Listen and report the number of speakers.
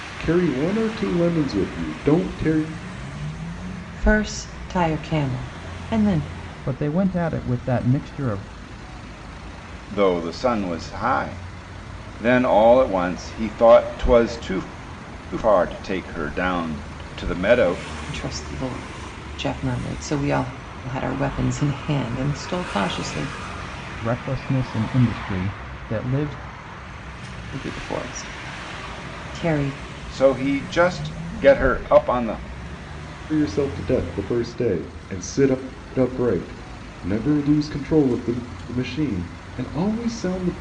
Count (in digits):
4